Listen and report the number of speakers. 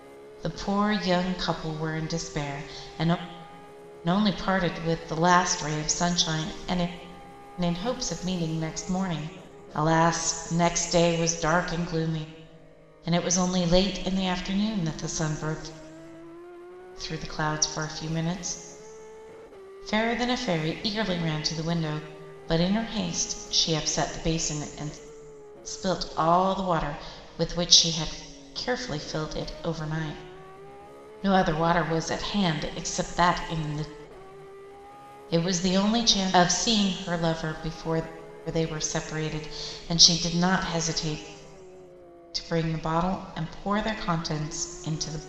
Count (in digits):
1